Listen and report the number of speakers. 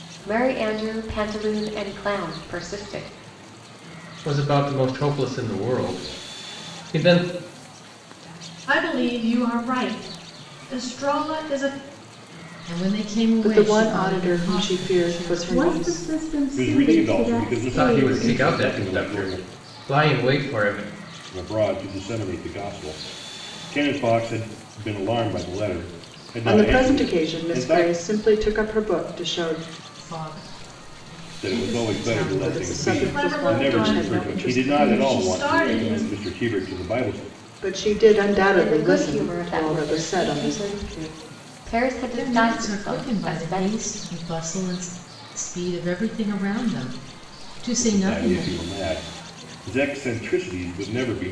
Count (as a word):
seven